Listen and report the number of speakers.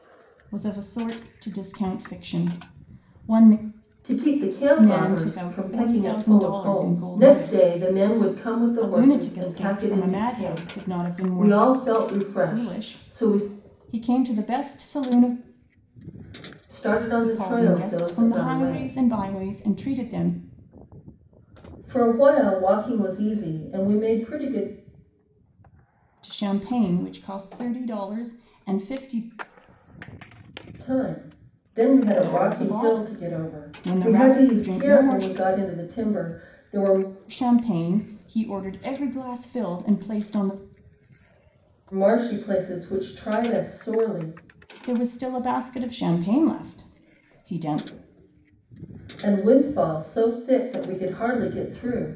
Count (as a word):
two